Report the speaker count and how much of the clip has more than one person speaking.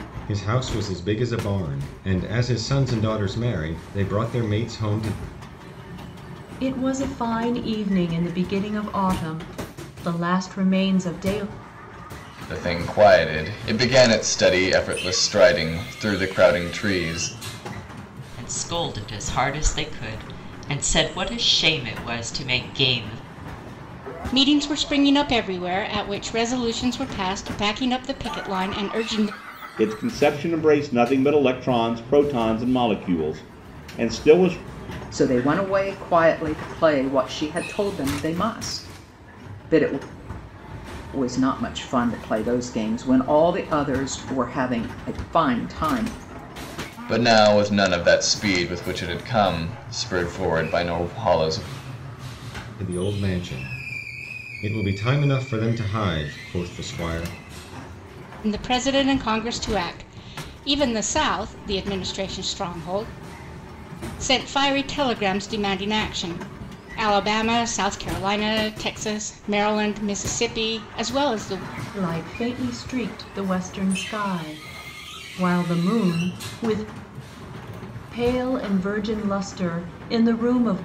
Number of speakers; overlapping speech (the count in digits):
7, no overlap